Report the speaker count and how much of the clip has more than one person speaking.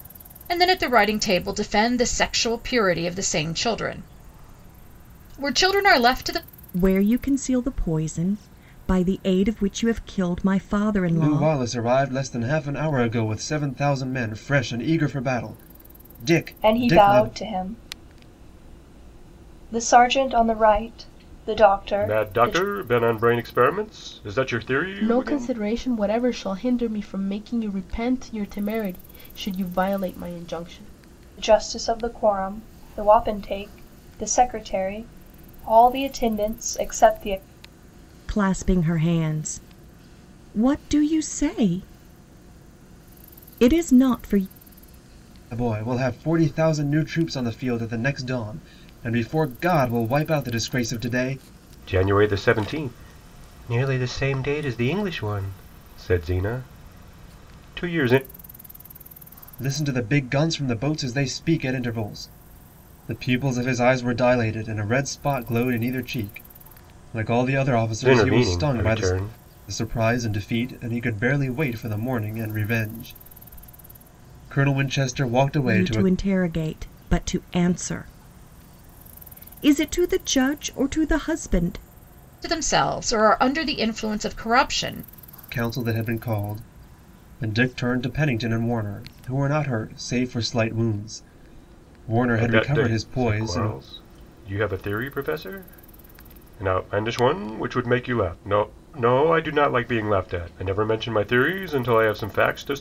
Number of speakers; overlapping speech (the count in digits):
6, about 5%